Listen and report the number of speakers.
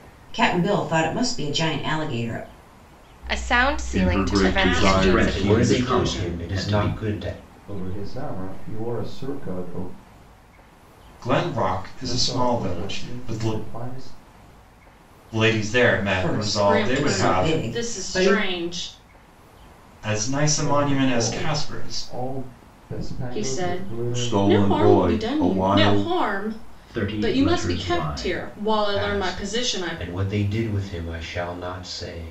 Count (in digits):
8